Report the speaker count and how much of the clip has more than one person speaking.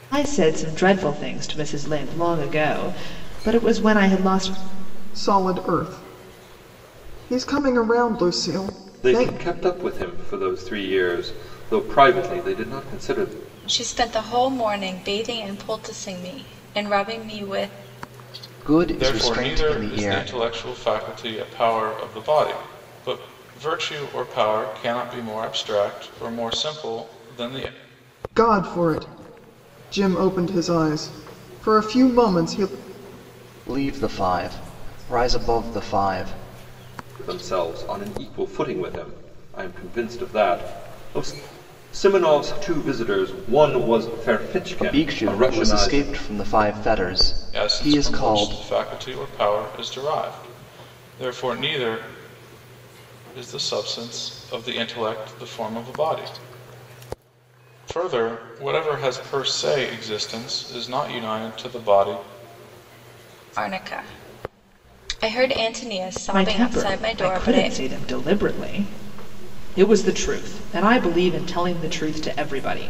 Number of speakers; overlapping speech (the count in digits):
6, about 8%